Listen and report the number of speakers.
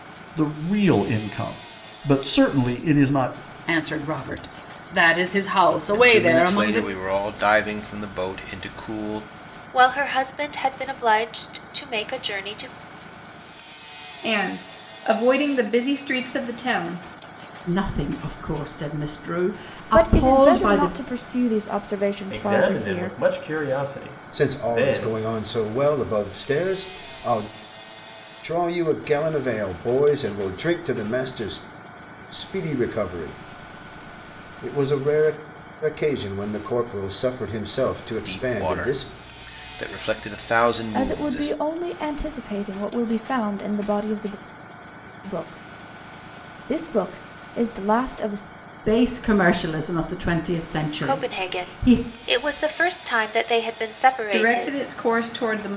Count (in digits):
9